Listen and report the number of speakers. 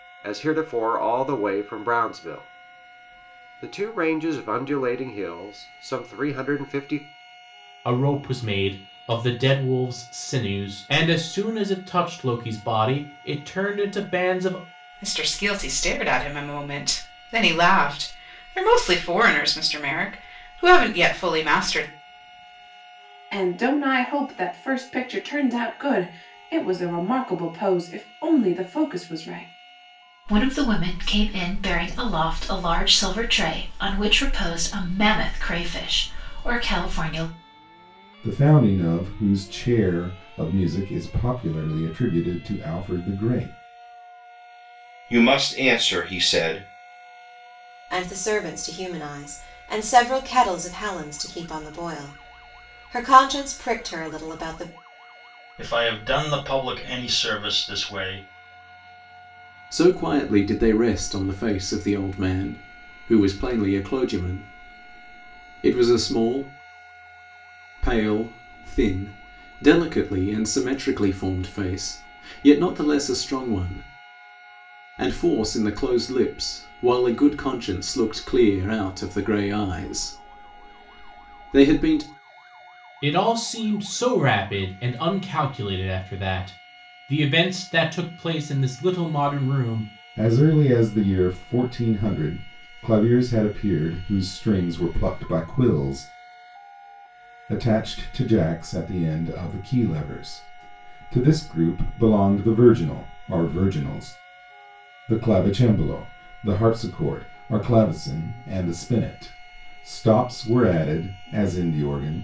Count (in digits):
10